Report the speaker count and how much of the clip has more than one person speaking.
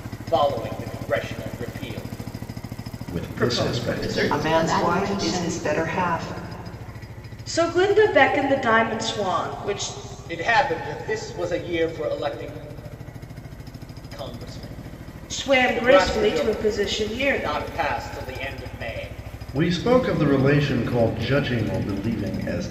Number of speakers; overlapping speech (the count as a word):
five, about 17%